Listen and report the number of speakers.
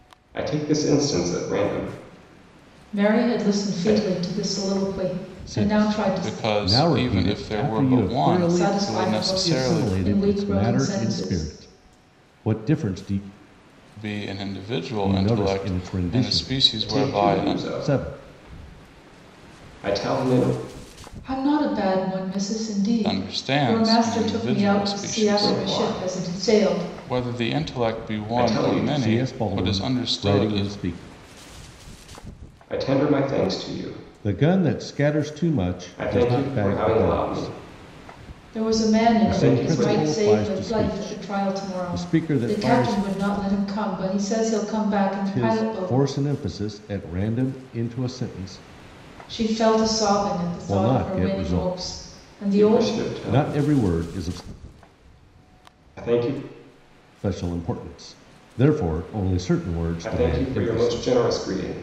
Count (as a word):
four